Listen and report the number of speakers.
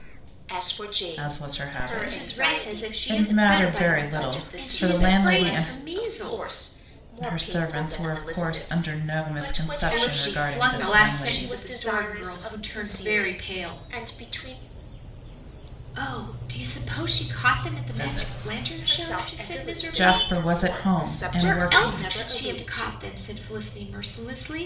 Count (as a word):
three